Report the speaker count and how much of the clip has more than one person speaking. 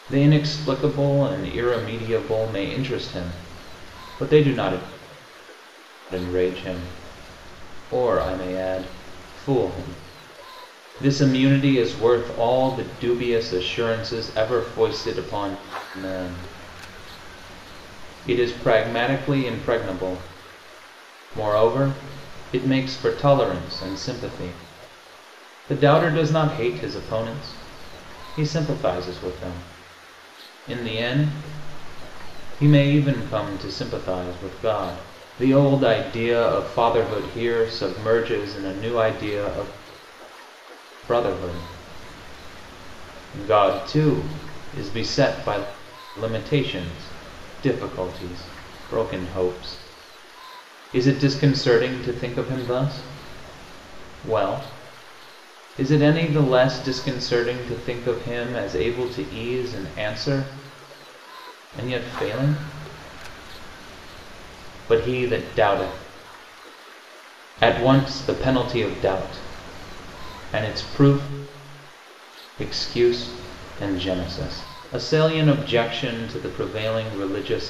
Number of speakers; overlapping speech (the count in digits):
1, no overlap